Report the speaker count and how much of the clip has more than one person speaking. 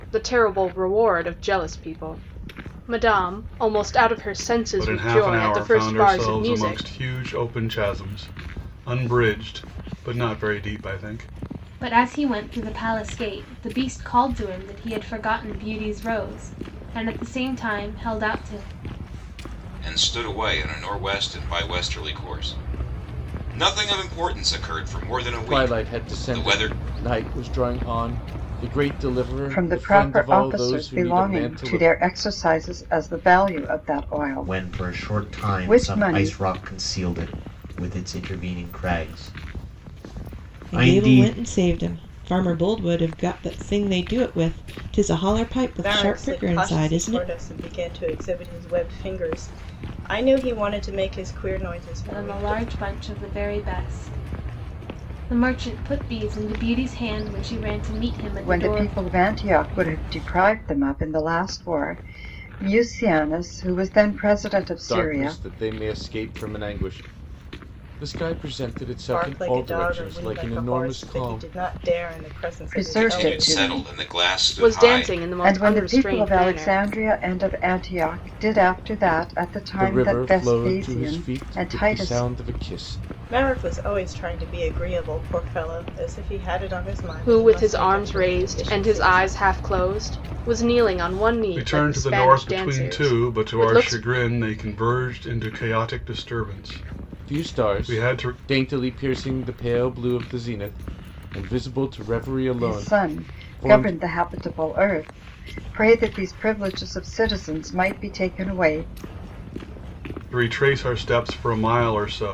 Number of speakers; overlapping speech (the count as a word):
nine, about 24%